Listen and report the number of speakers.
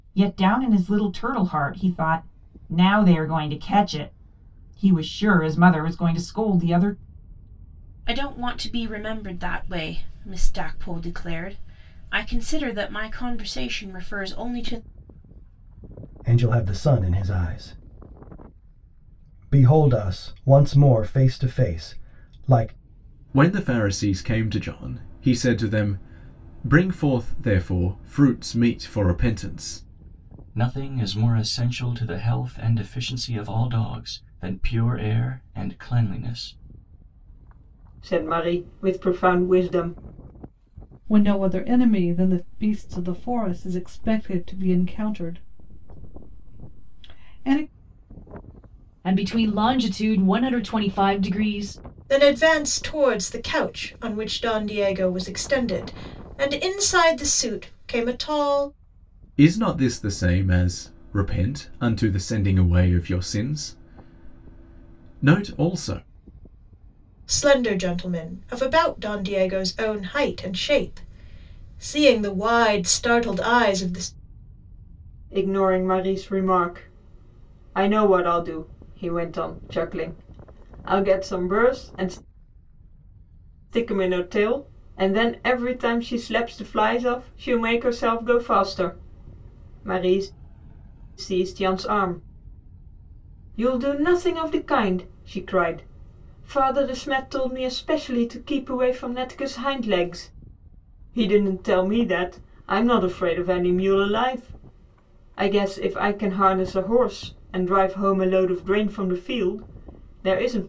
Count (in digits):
9